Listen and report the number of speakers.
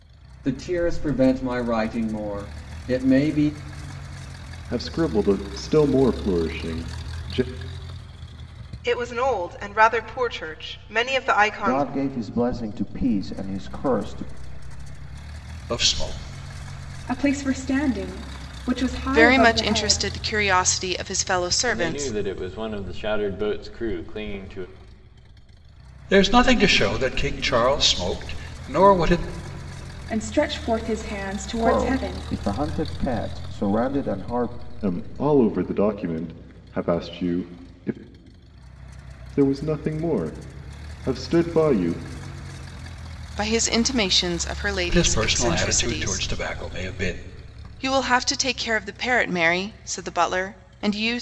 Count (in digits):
8